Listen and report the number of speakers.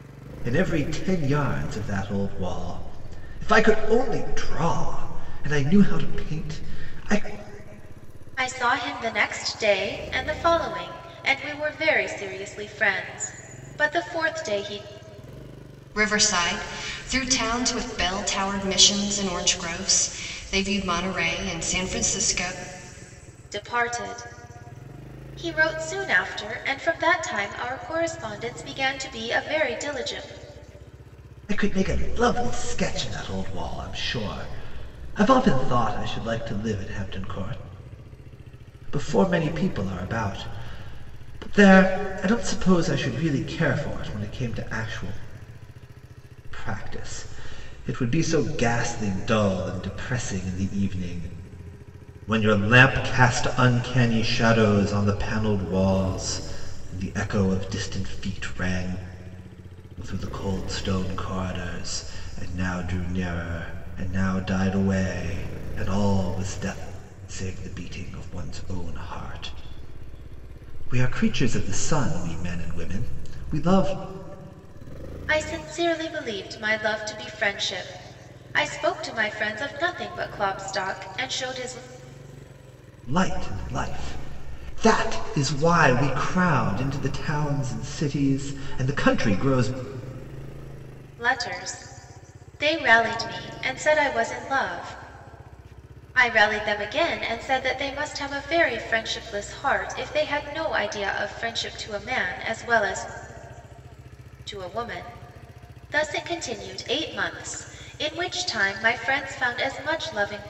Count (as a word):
three